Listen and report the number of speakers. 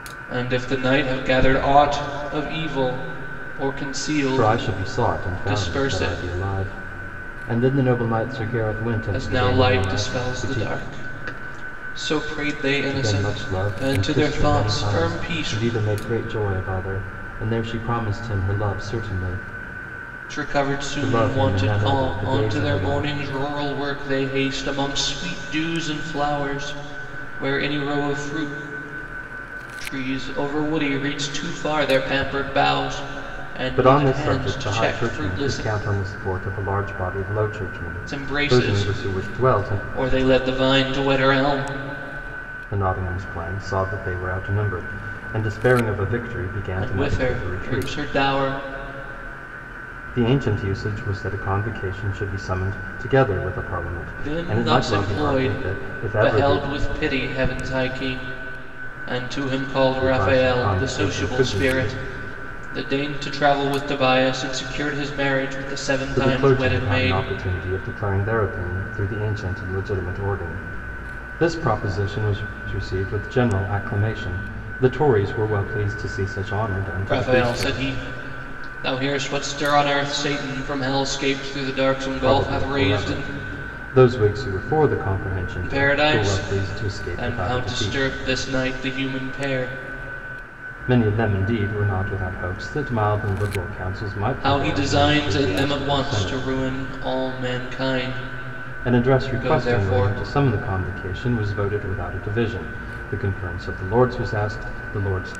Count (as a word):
two